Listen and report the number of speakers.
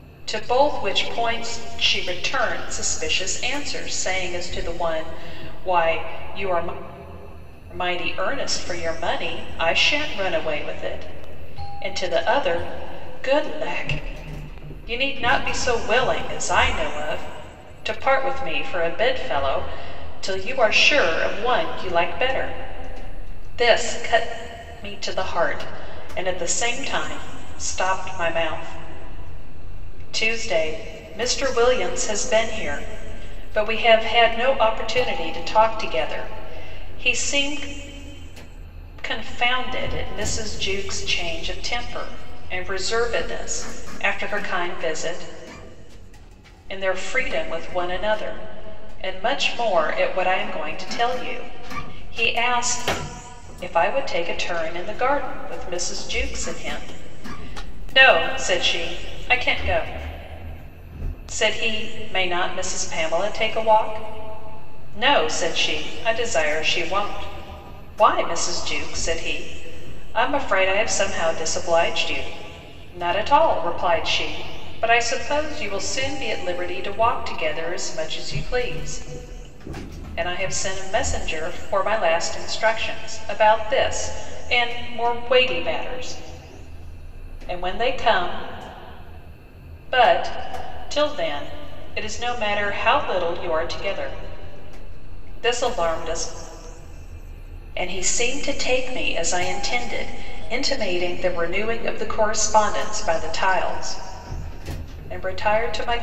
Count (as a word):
one